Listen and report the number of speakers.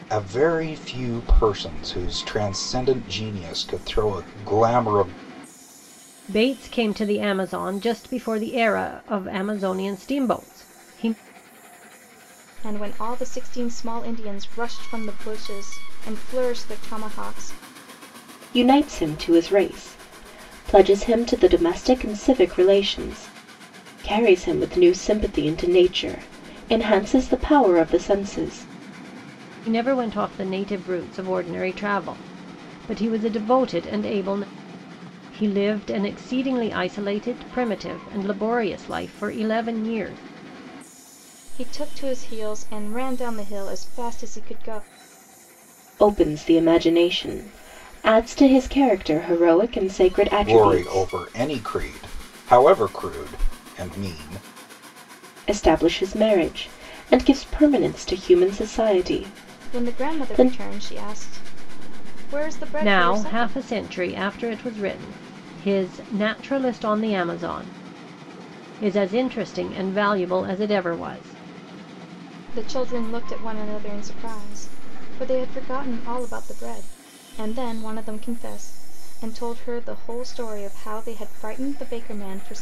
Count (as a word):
four